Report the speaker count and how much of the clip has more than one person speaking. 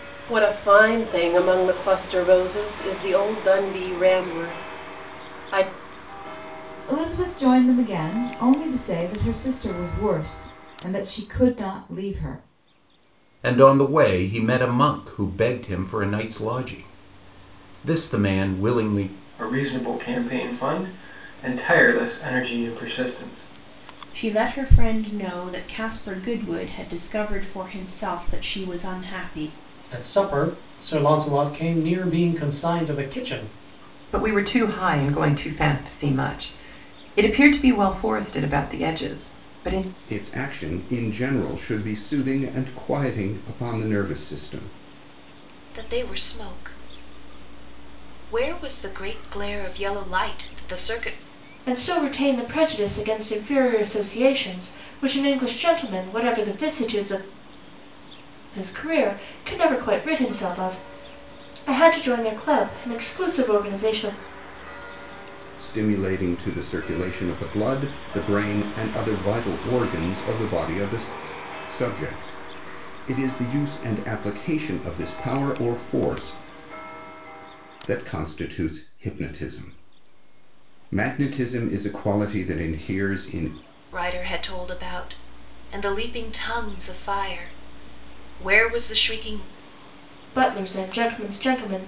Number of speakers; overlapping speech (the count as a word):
ten, no overlap